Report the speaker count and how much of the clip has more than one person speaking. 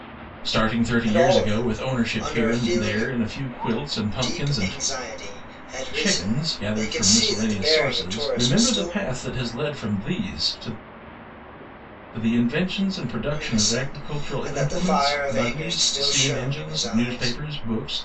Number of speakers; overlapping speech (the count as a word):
two, about 54%